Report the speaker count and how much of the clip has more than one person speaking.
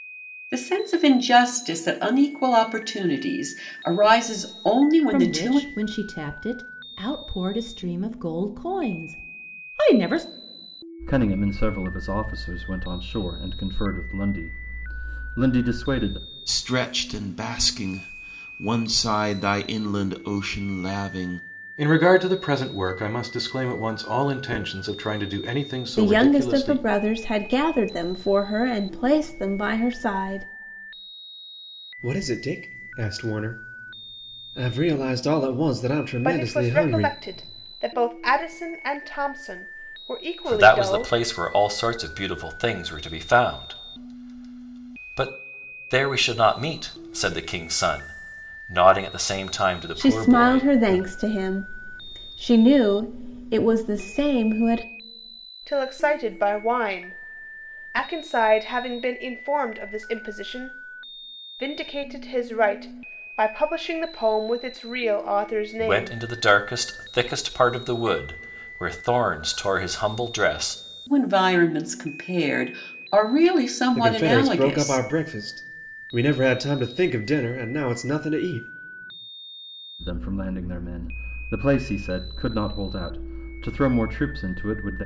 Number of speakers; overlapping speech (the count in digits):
9, about 7%